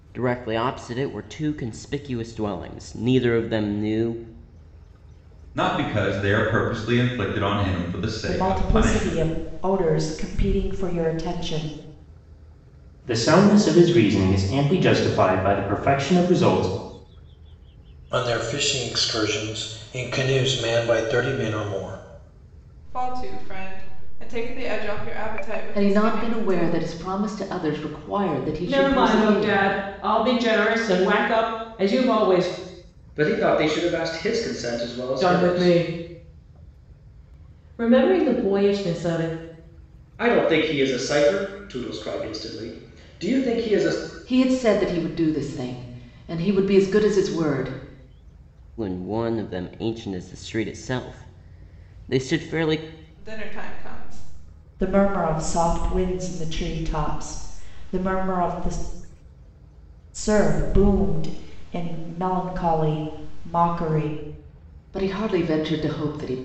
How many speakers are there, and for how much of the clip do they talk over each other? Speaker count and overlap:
9, about 6%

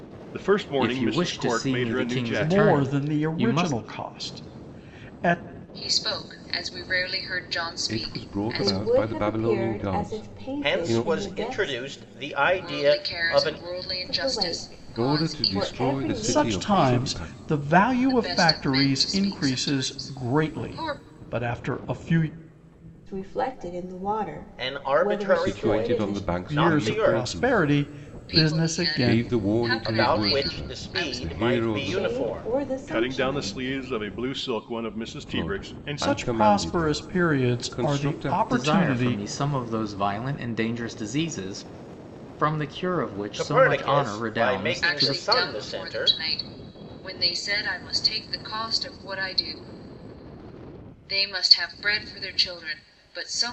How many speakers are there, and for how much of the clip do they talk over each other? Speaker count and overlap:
7, about 57%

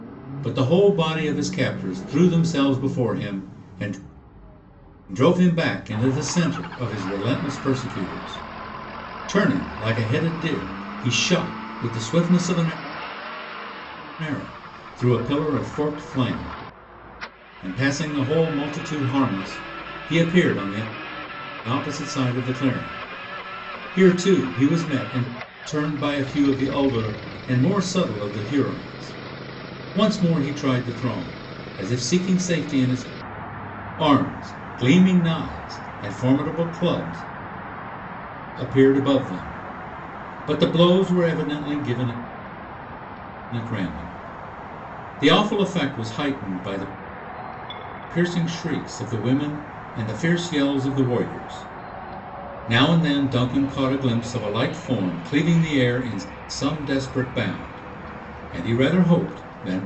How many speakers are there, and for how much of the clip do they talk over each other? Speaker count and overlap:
1, no overlap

